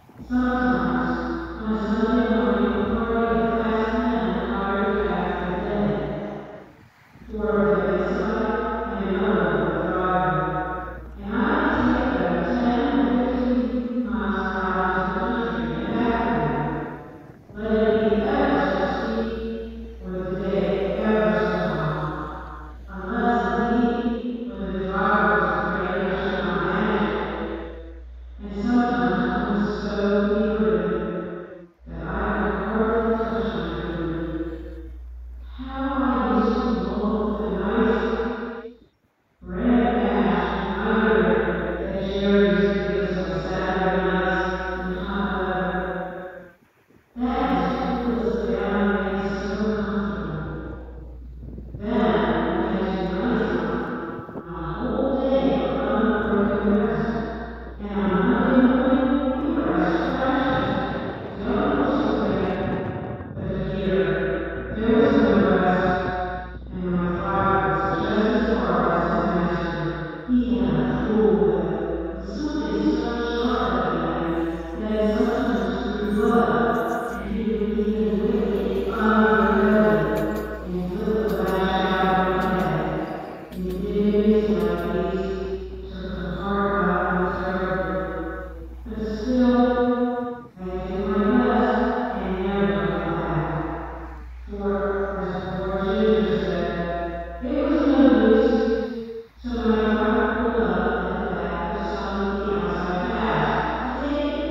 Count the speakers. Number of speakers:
1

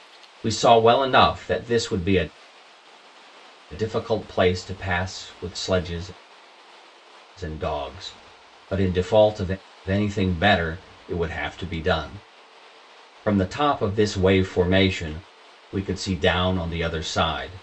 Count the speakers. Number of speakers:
1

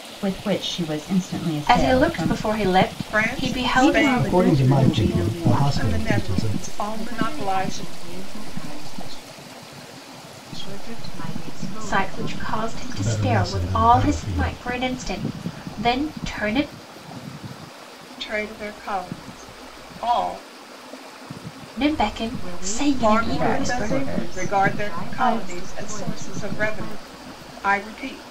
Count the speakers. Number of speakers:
6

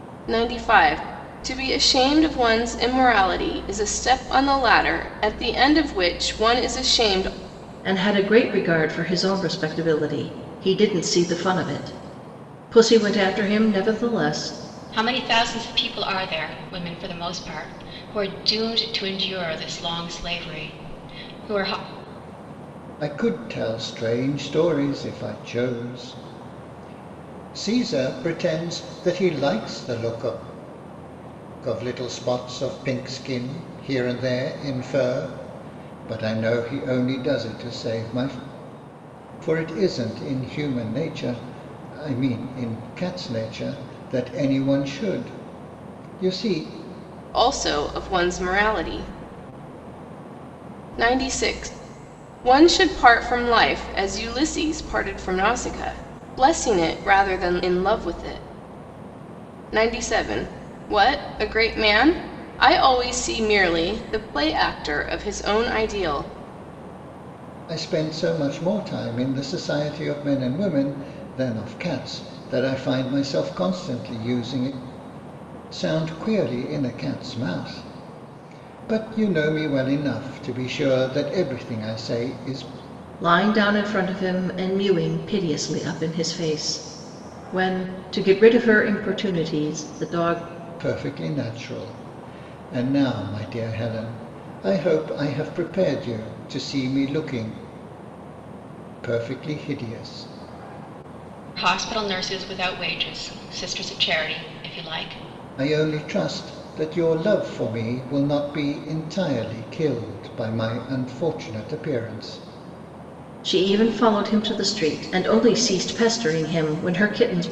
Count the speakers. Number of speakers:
4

